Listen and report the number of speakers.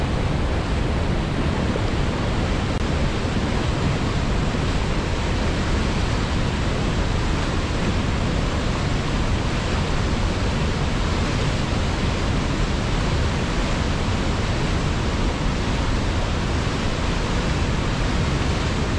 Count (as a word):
zero